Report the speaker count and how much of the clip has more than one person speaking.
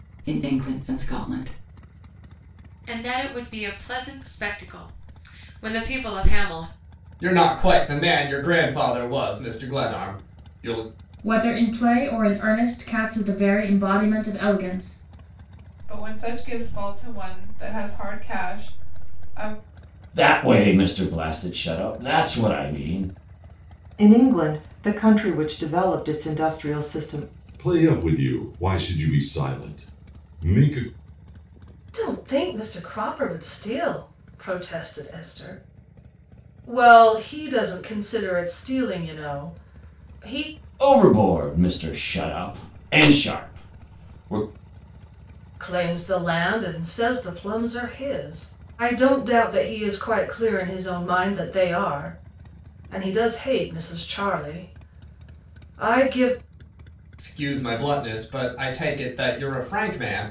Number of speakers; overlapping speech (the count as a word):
nine, no overlap